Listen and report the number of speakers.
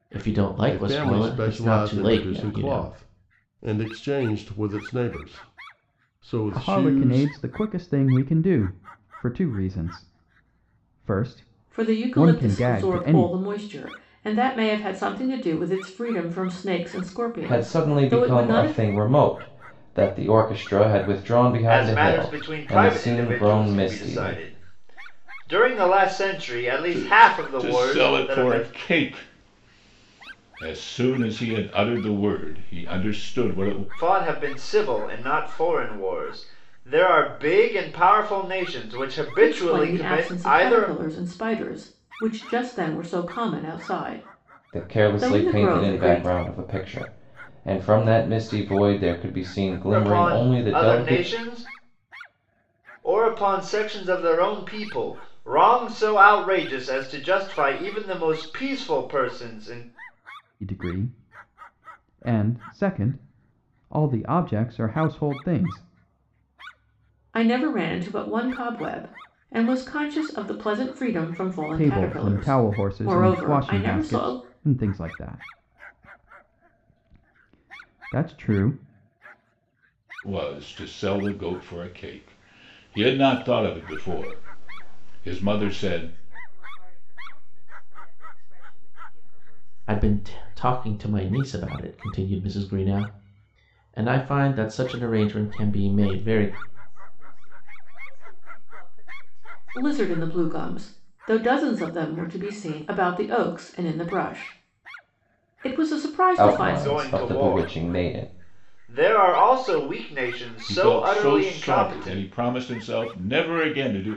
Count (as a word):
eight